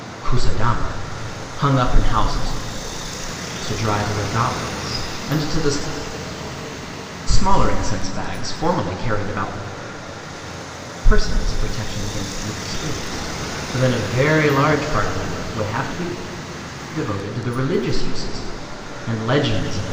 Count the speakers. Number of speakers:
1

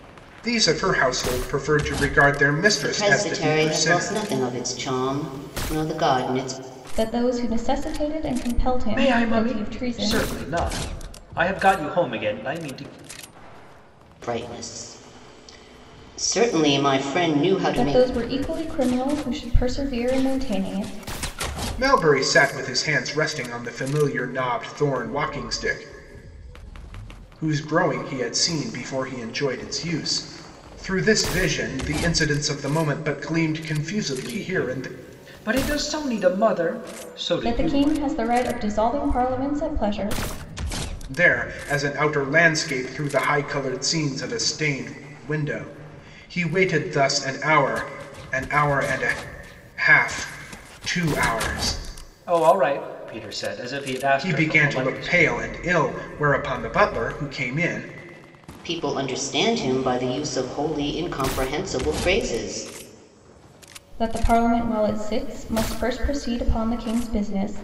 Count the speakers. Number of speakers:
4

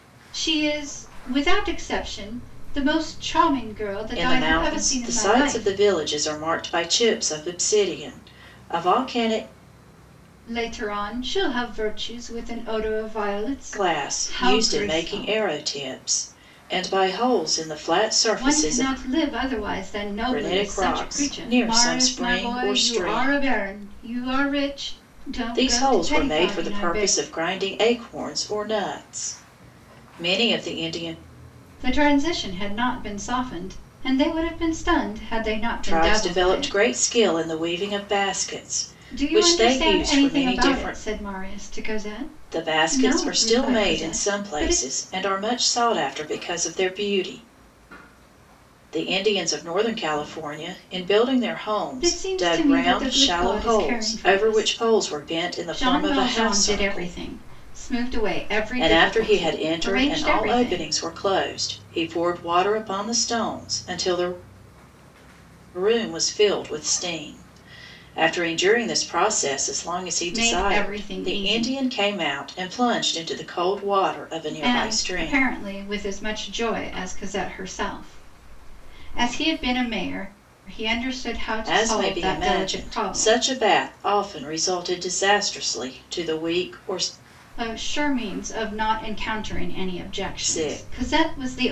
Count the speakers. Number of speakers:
2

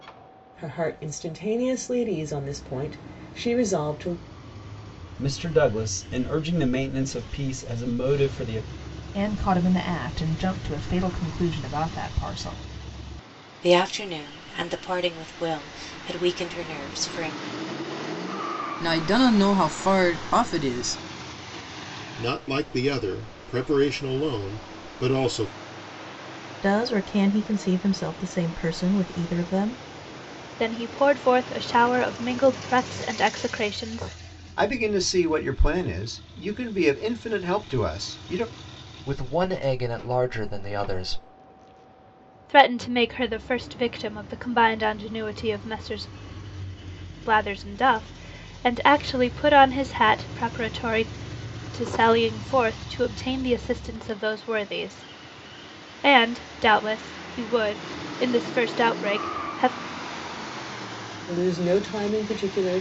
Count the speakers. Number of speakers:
10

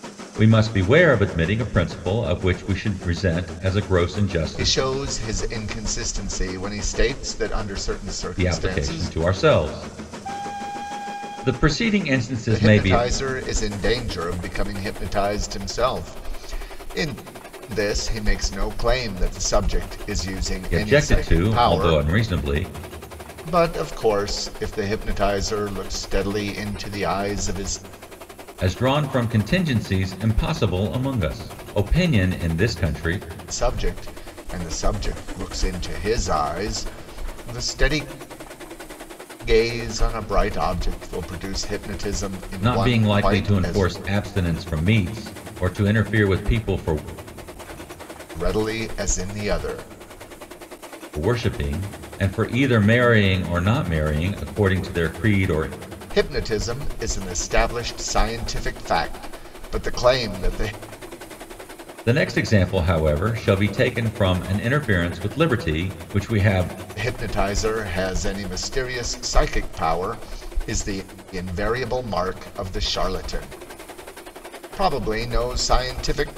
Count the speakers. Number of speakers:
2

